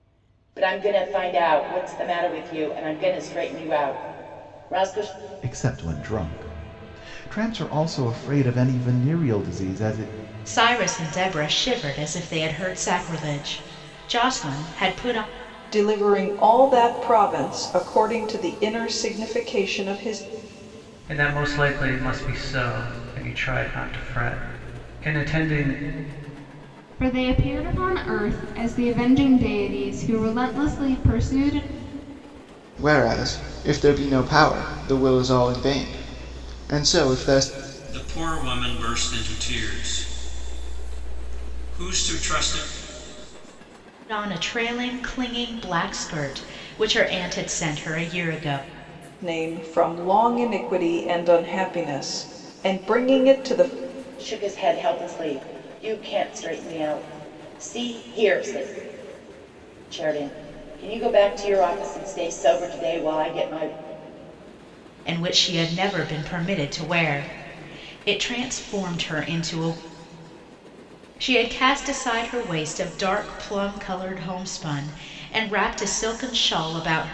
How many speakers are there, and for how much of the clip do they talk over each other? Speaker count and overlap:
8, no overlap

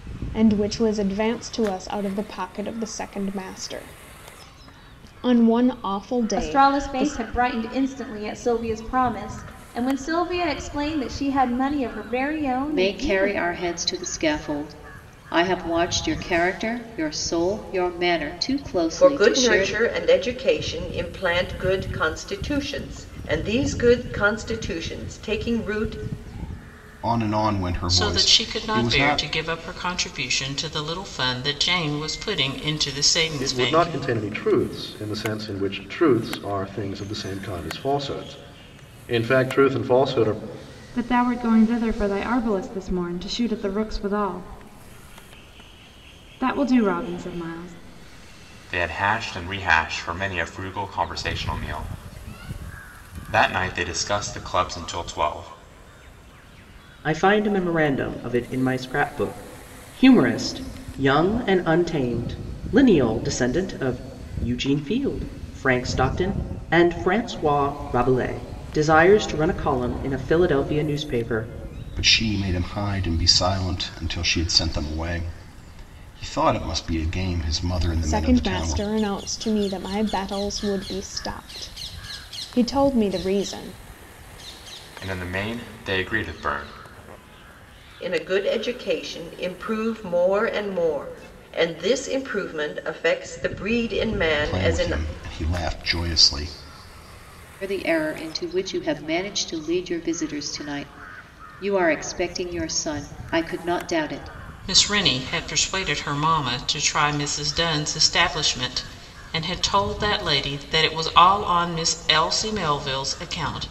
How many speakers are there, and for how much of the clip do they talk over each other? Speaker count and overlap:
10, about 5%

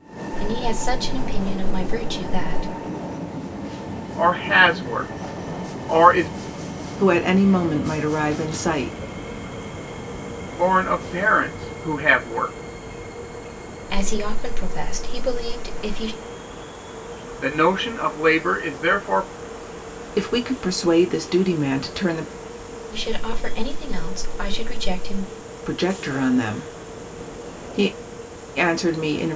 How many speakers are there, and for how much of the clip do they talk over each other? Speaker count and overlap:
3, no overlap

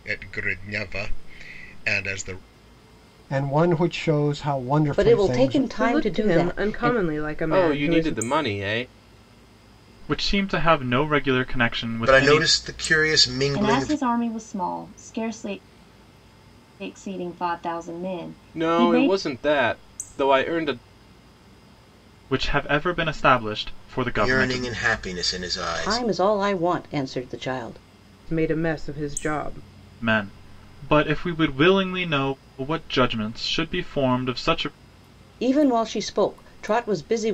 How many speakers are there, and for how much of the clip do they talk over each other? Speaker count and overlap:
8, about 14%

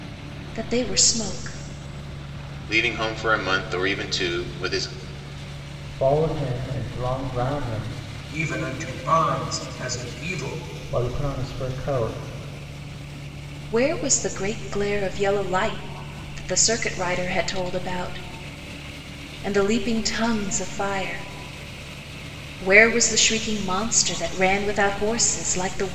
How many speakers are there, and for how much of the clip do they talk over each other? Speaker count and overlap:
4, no overlap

